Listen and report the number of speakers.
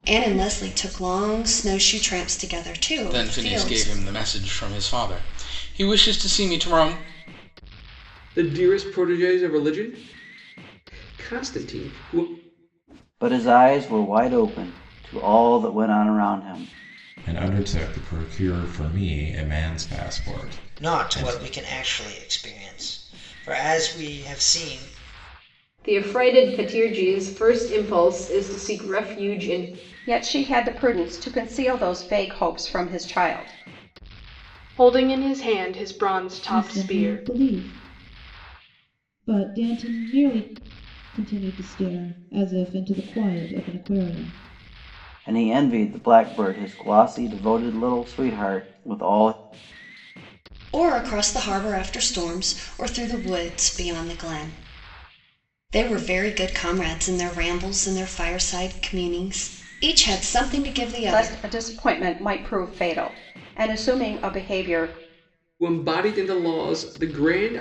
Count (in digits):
10